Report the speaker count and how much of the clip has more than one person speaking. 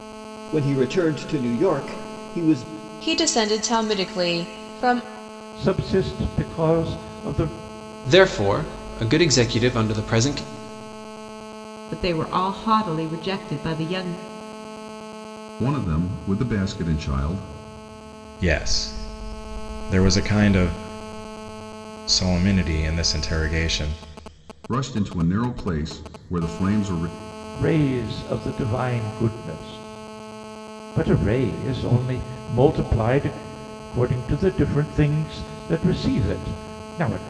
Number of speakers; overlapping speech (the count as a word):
seven, no overlap